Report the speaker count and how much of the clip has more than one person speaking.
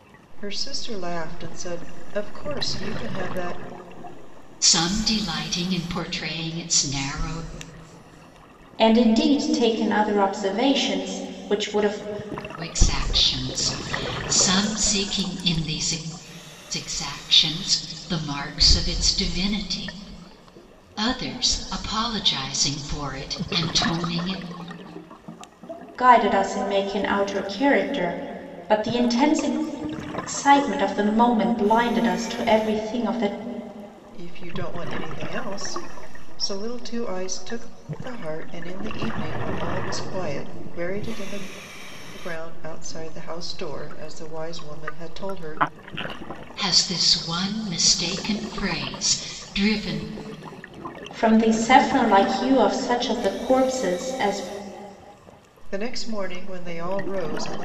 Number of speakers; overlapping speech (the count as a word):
three, no overlap